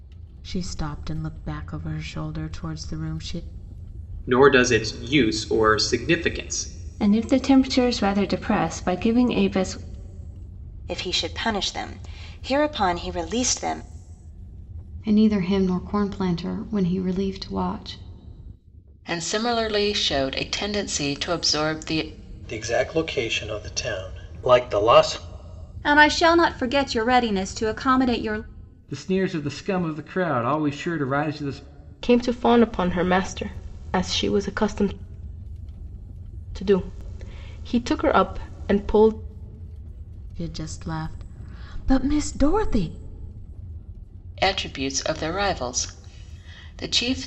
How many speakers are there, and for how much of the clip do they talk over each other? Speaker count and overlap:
10, no overlap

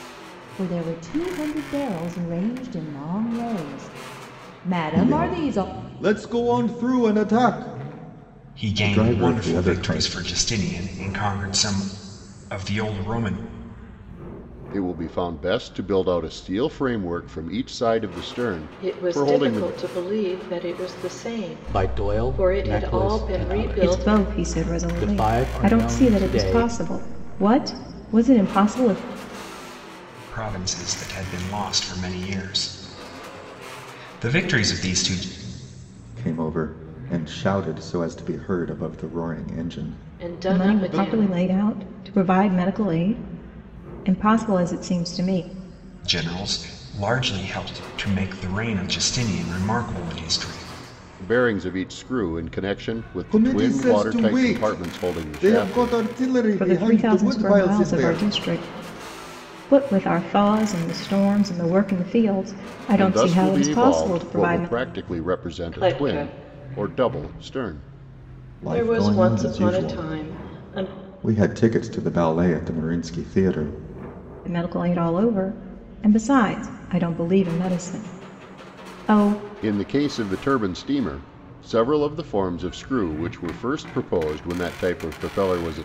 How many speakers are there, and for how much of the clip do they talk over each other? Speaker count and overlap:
7, about 24%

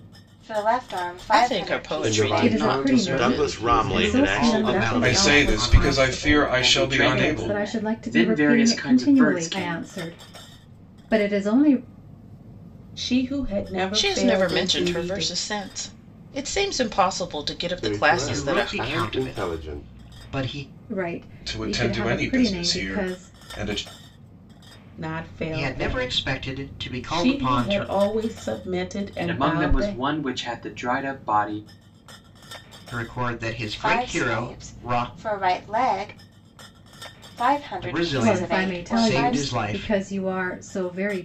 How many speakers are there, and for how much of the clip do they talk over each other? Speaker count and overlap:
9, about 51%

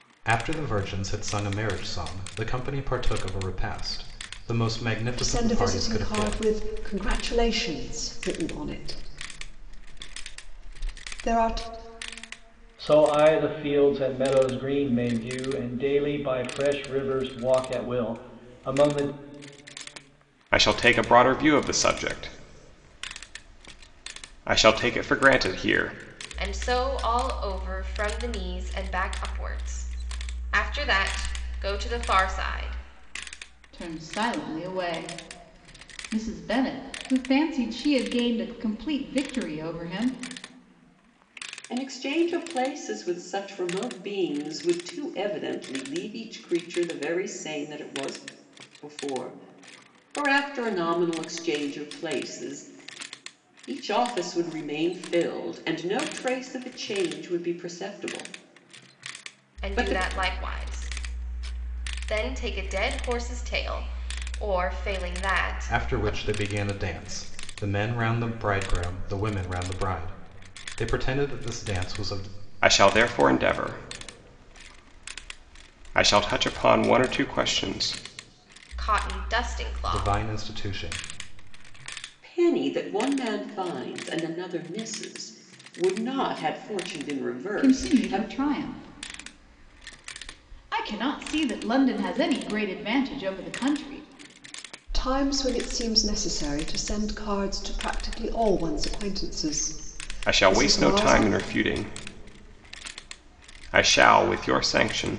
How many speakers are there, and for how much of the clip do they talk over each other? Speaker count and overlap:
7, about 4%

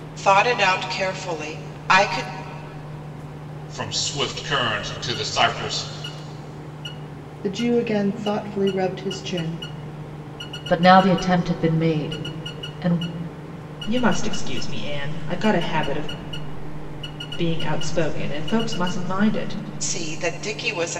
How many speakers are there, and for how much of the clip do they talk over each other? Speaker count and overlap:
5, no overlap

